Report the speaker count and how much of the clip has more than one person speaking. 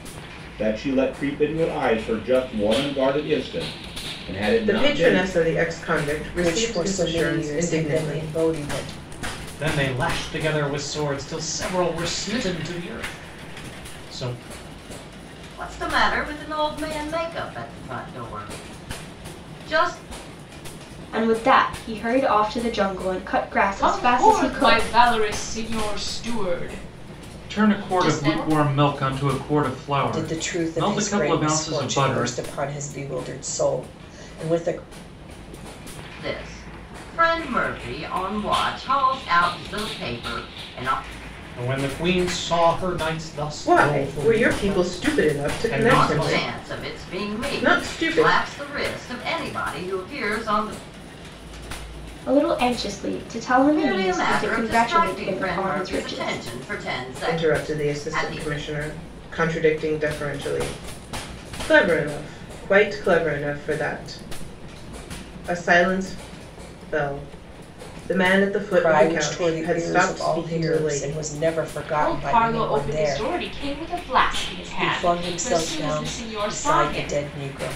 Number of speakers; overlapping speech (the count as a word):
eight, about 28%